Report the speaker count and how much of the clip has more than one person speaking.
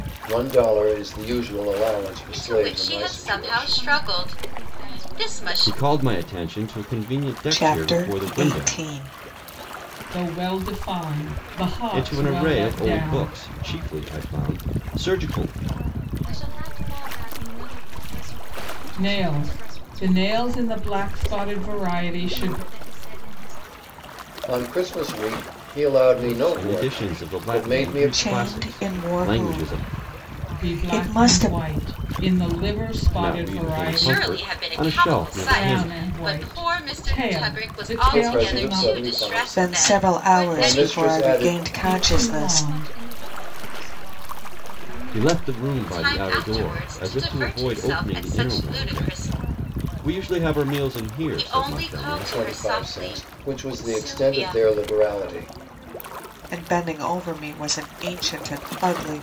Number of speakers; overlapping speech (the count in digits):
6, about 54%